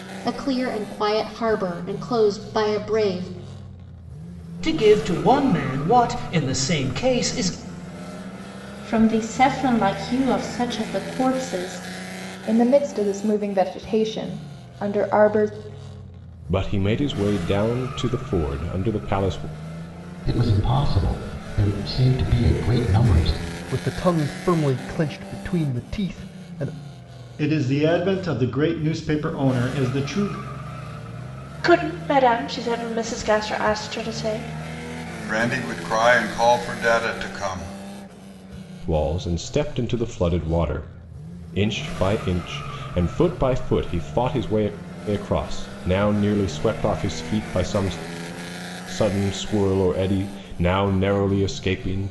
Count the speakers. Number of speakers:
ten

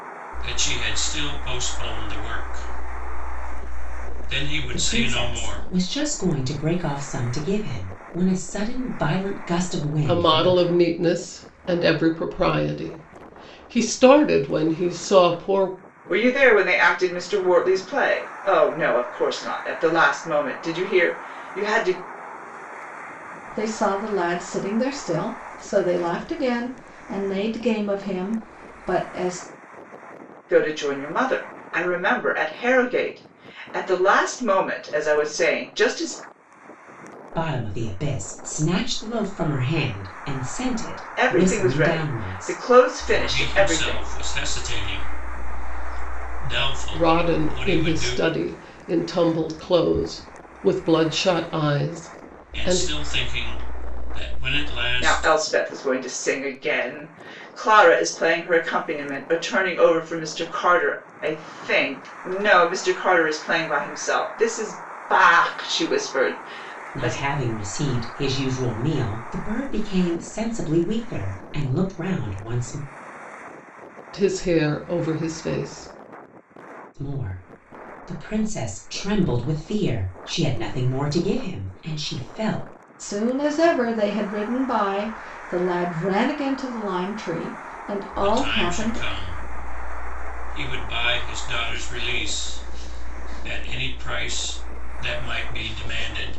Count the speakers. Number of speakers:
five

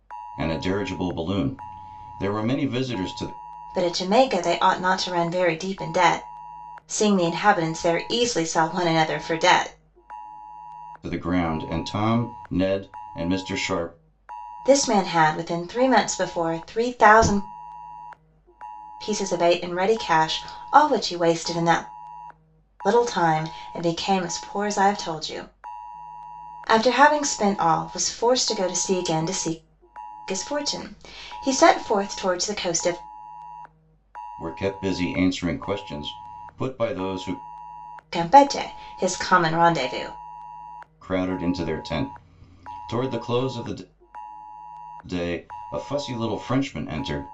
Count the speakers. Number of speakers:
two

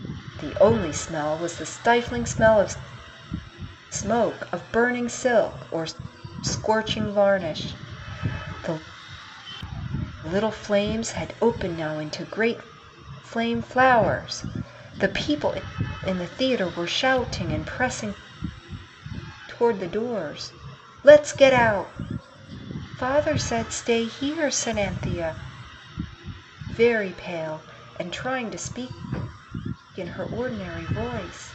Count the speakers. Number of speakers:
one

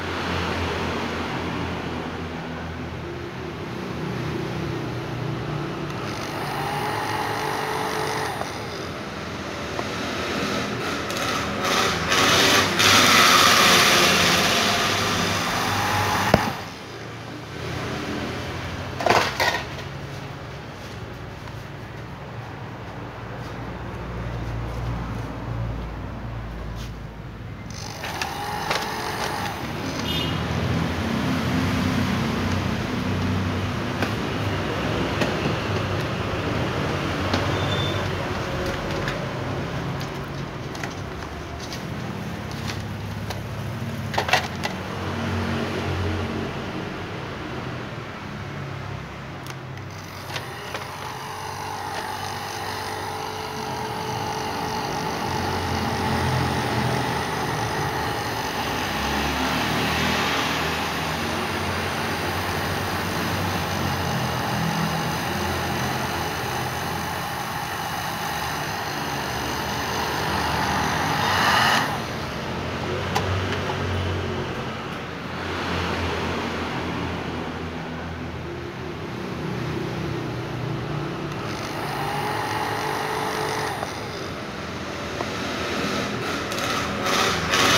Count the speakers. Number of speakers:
zero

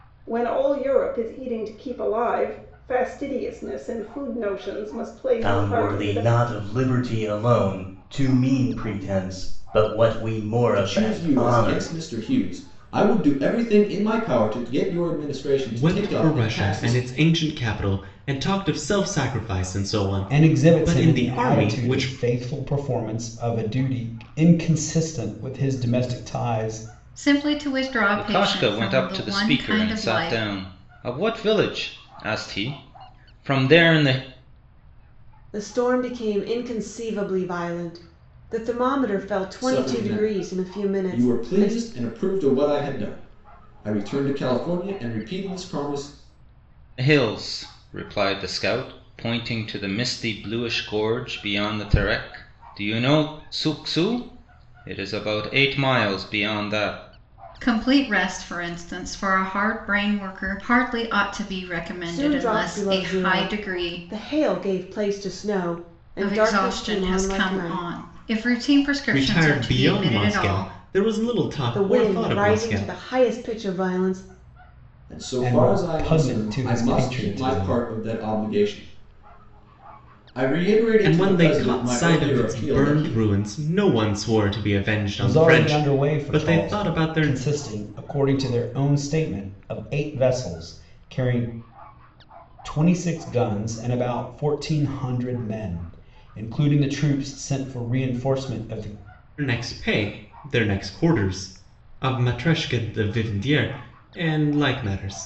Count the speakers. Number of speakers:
eight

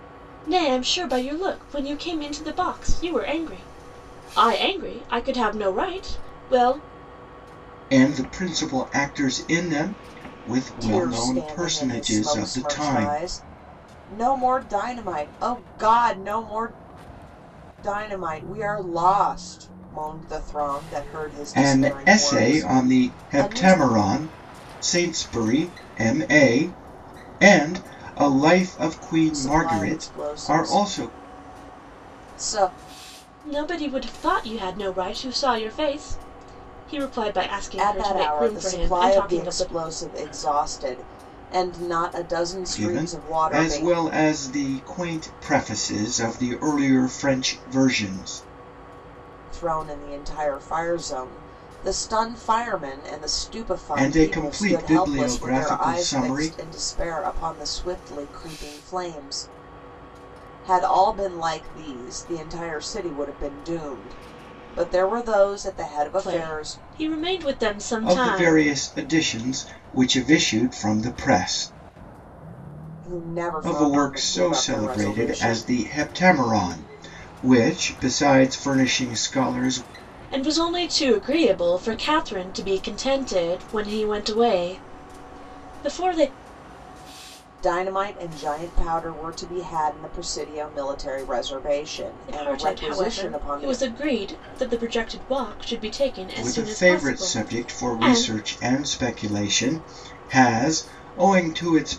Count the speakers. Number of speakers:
three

